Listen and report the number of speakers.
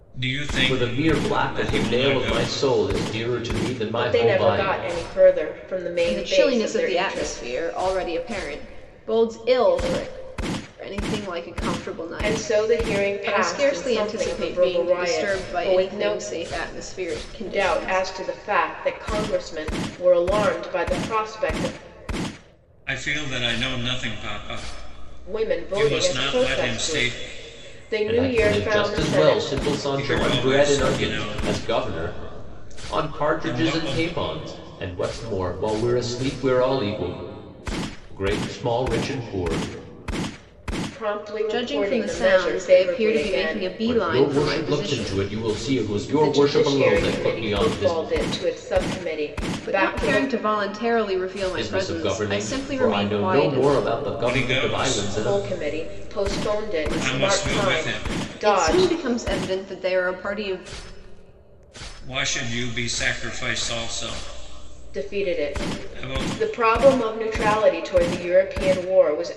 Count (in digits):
4